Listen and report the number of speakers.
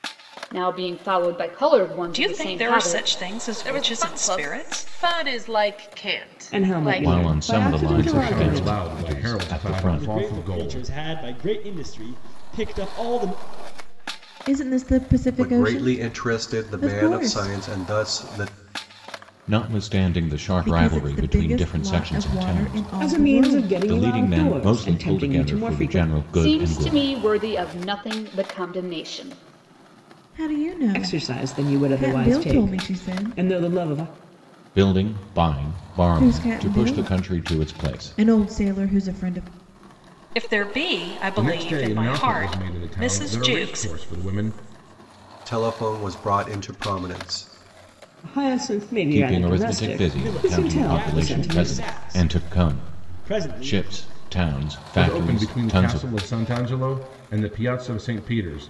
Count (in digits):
9